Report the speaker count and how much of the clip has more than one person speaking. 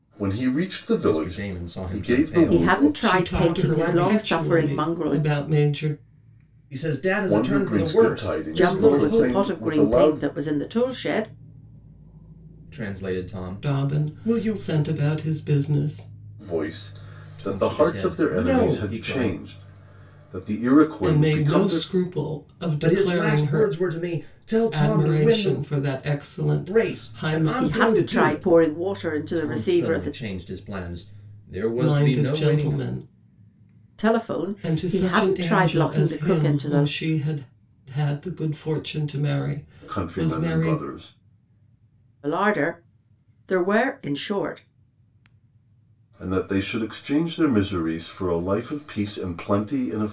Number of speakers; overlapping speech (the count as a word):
four, about 42%